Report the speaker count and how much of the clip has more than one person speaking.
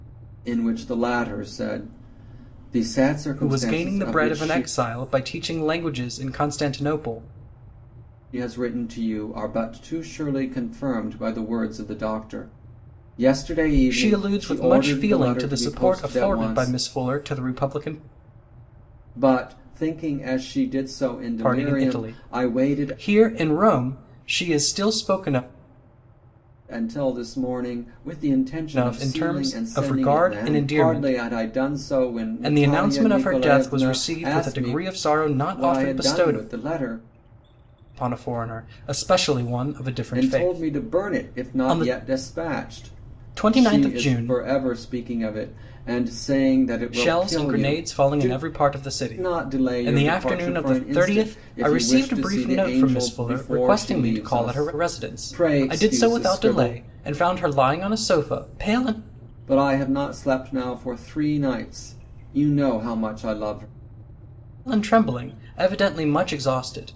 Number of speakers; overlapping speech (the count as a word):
two, about 35%